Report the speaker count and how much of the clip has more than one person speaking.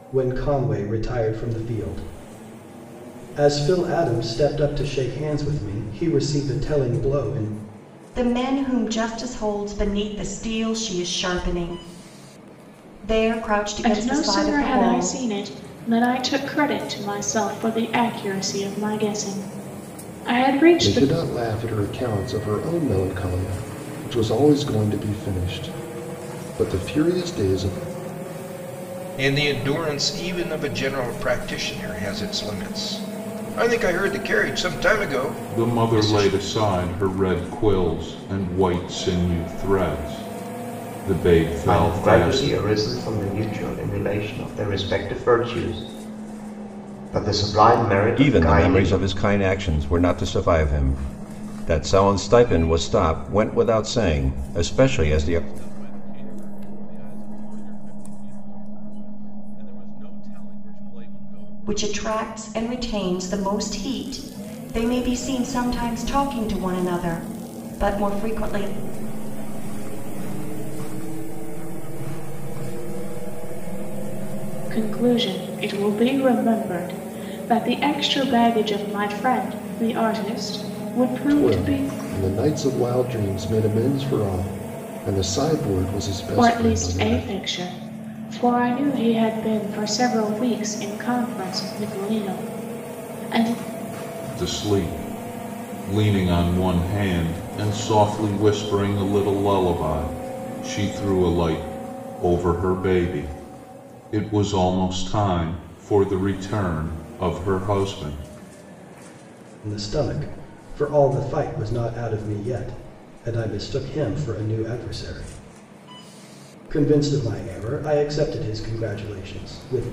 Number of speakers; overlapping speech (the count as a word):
nine, about 7%